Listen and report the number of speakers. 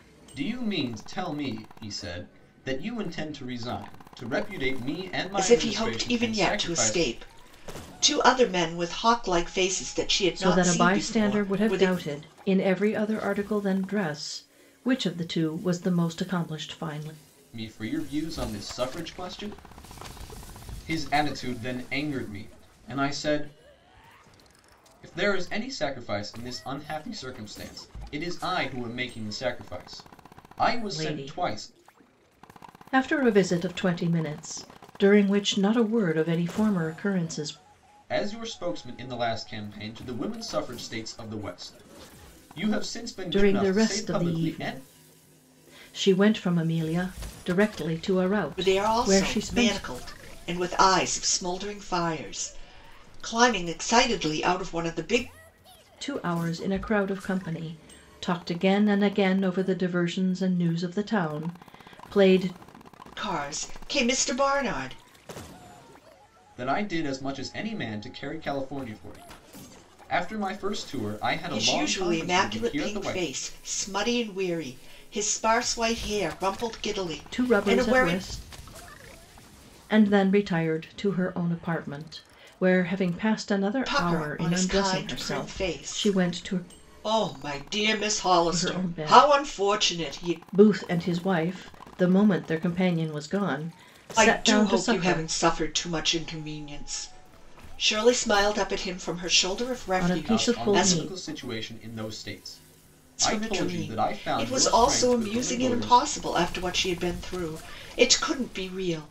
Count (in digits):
3